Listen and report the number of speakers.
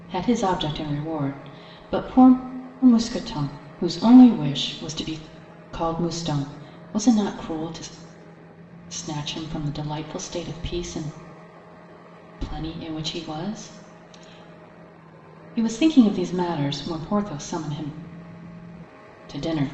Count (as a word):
one